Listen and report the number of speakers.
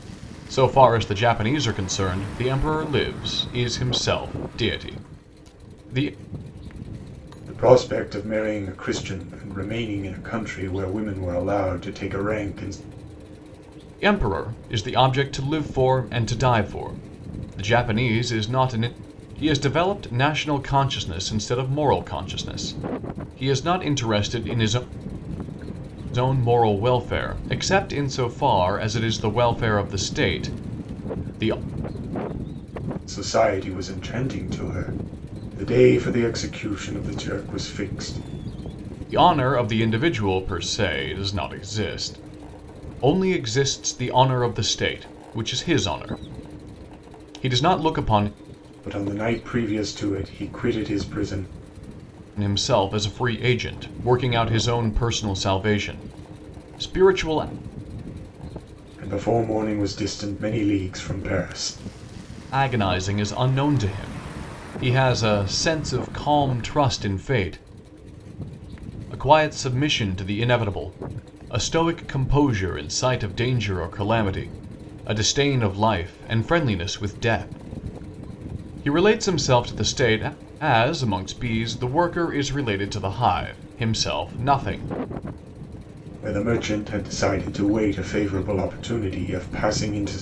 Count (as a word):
two